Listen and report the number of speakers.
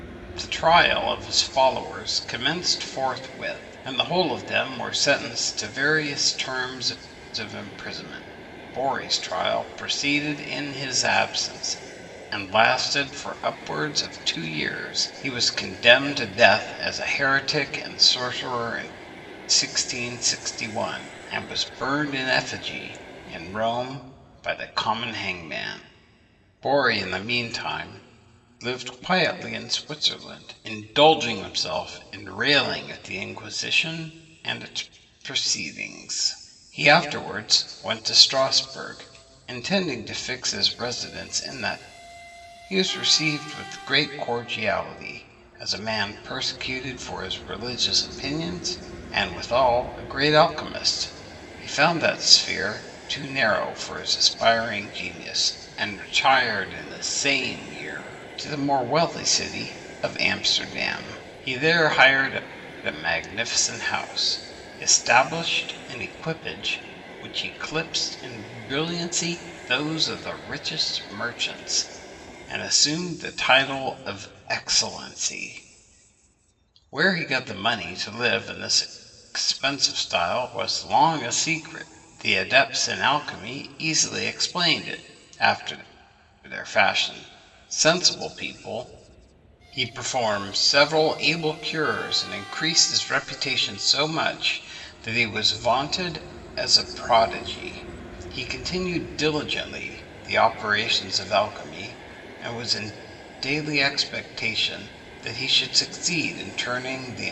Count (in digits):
1